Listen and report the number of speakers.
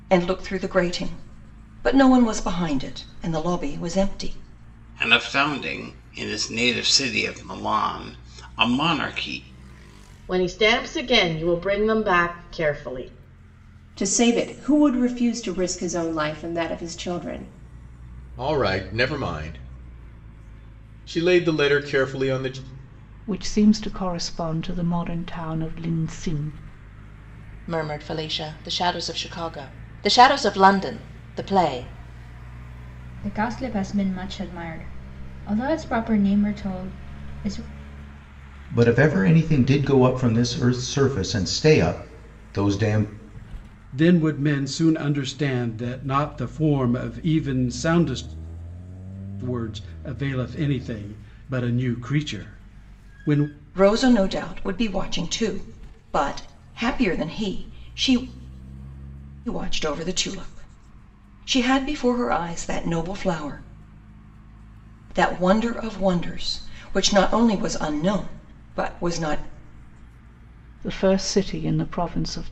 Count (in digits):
10